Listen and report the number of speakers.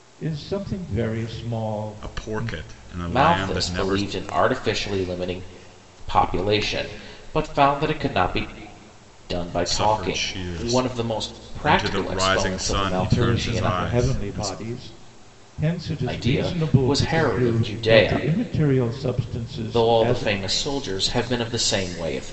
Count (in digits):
3